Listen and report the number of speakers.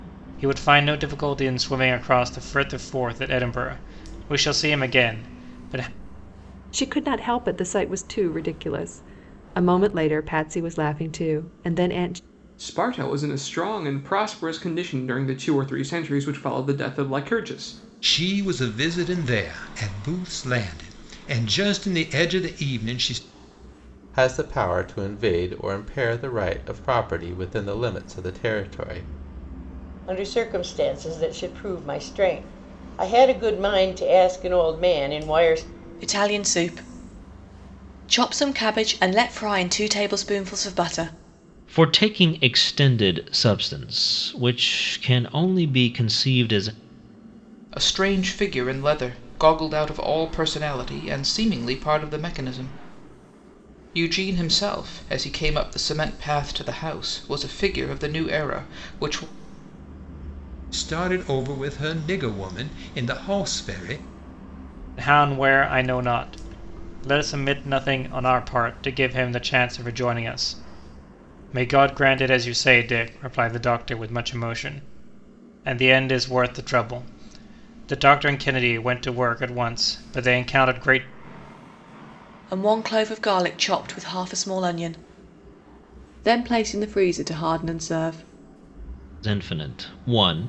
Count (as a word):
nine